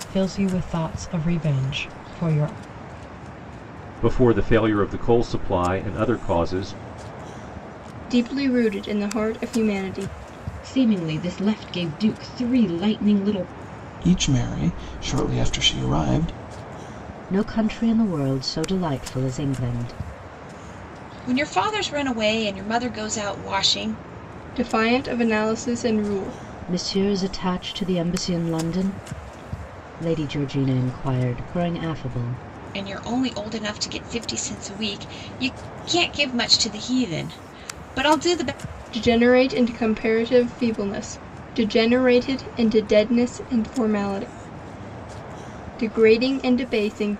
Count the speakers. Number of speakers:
7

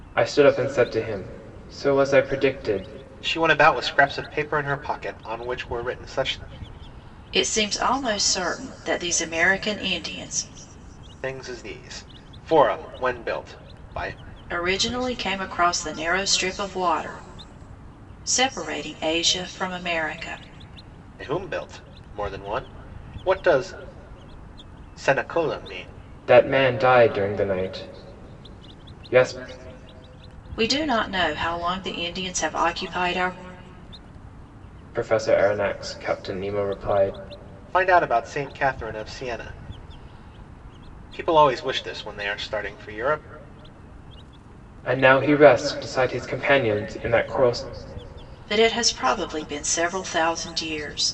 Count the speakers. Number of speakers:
3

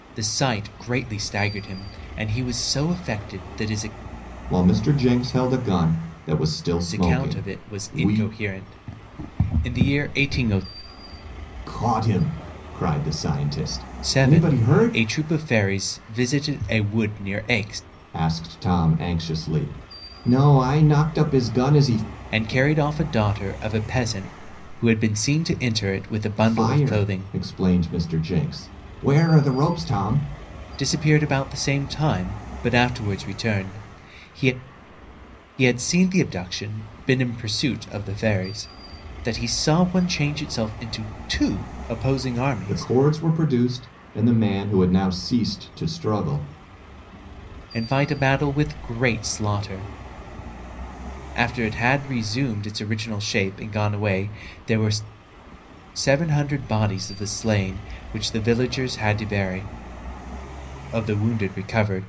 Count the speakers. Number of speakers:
2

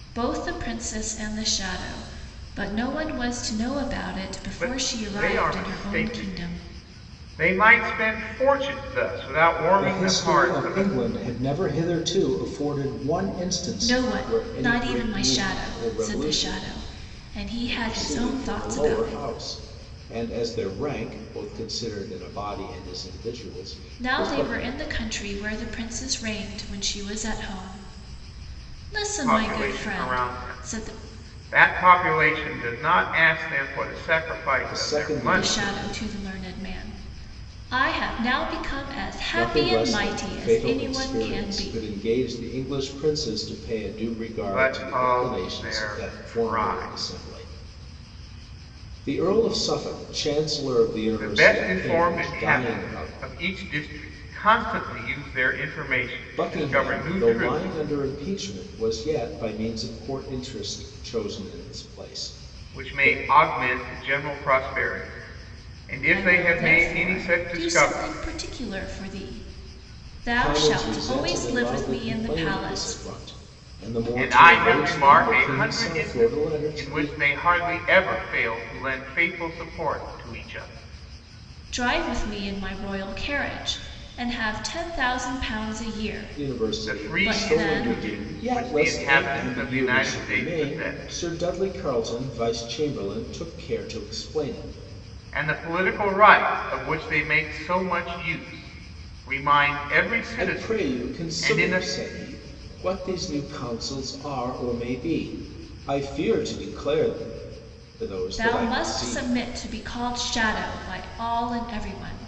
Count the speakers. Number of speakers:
3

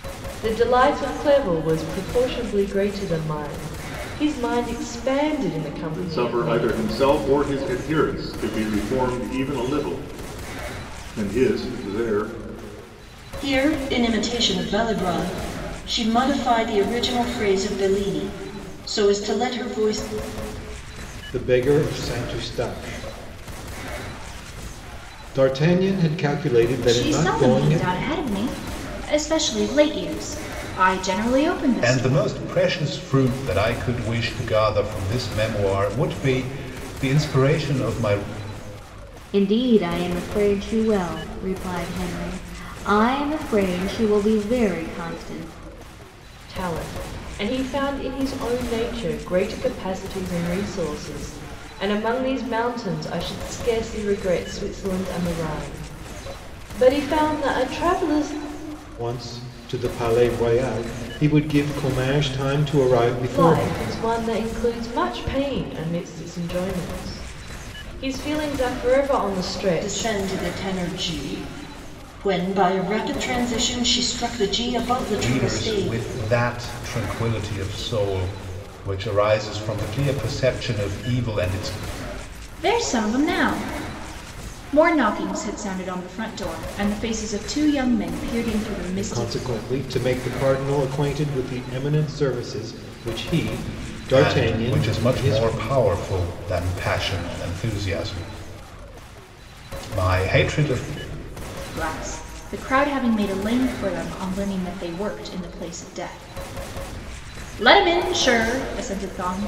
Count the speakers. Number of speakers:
7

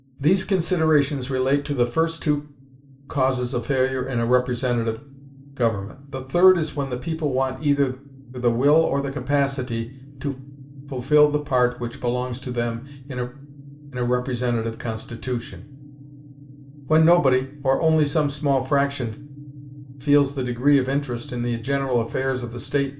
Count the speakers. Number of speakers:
1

